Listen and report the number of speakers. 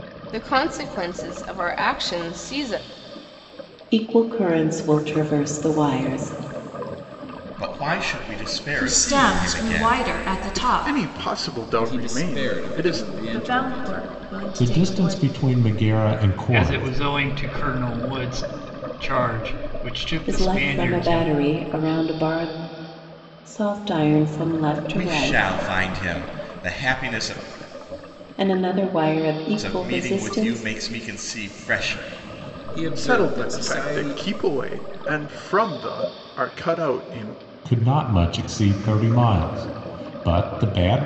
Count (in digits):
9